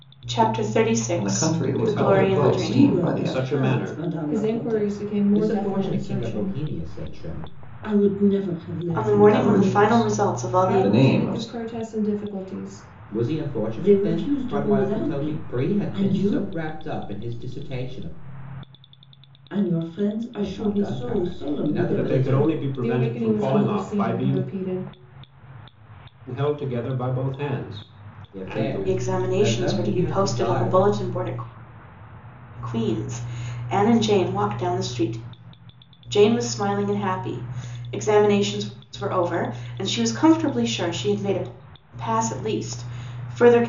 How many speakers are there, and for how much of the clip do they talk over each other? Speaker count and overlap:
six, about 38%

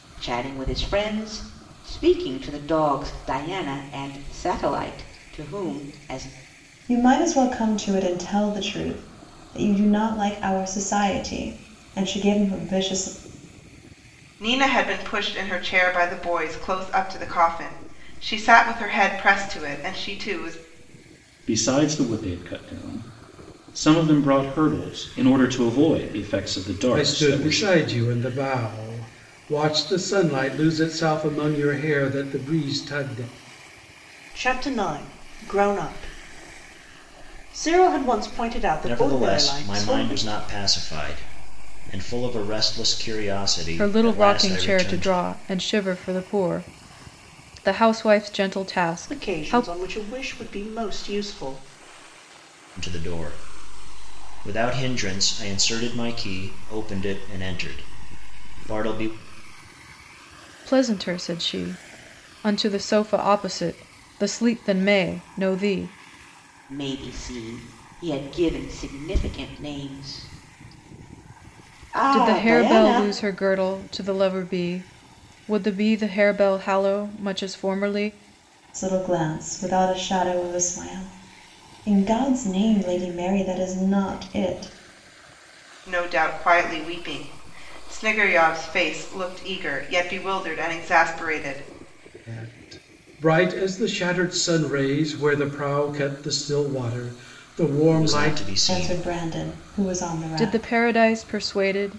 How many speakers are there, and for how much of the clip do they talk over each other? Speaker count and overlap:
eight, about 6%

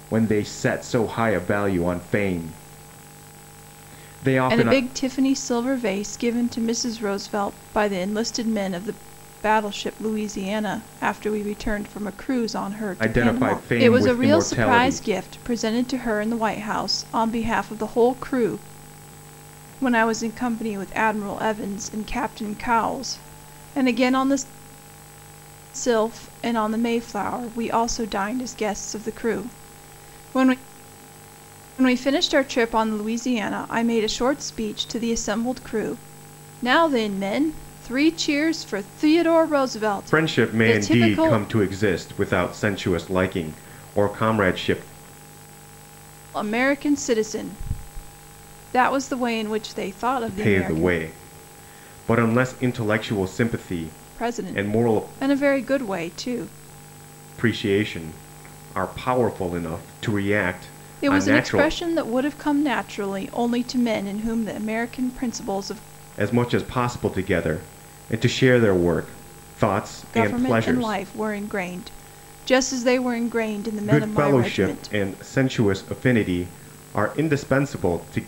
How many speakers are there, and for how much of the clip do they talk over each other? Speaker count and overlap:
two, about 10%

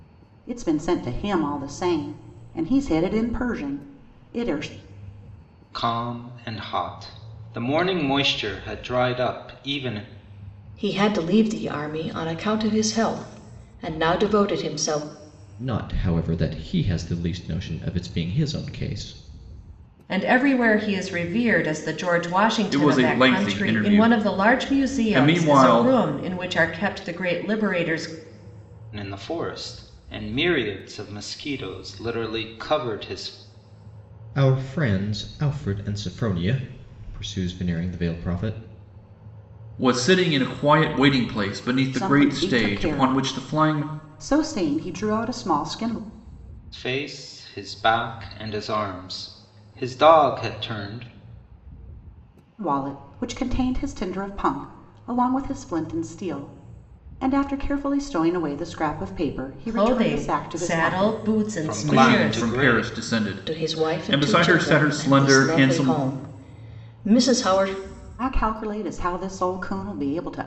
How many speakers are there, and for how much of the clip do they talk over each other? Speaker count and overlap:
six, about 15%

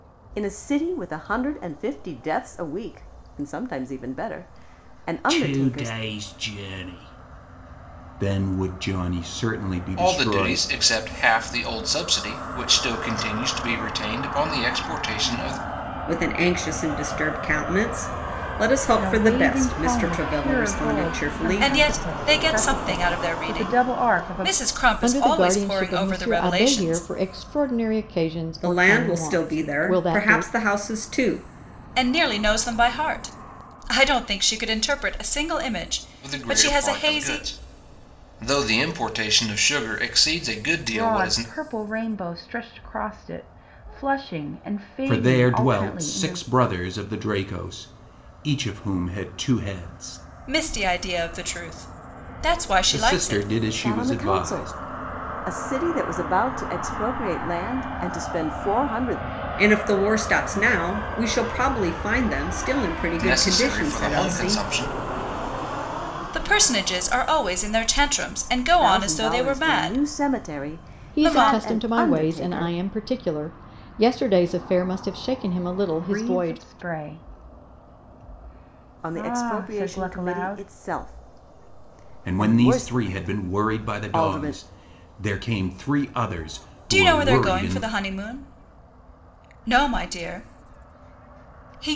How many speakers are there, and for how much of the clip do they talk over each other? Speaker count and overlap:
seven, about 30%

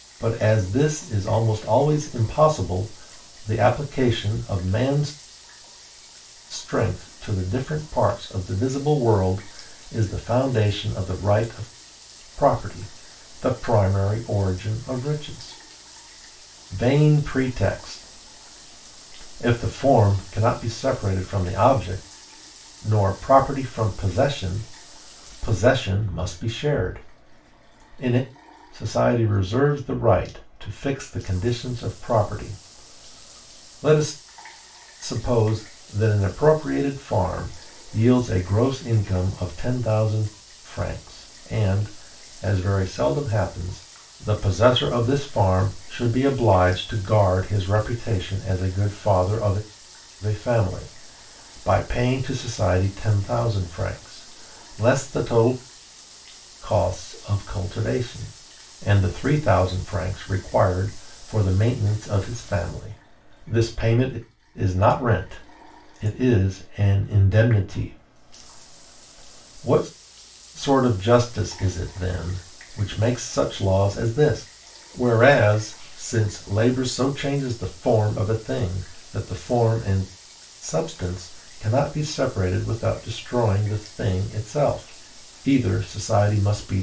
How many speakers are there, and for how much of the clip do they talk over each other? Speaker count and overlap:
one, no overlap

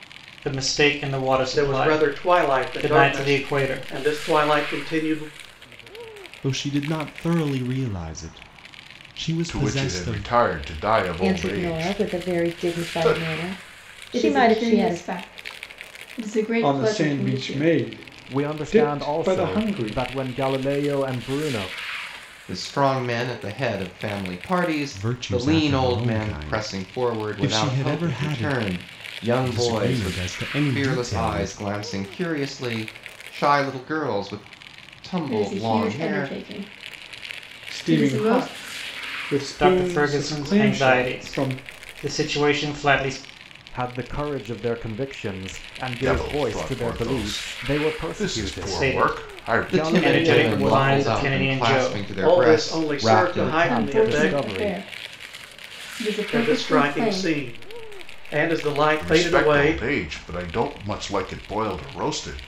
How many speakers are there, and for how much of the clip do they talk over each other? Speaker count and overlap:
nine, about 47%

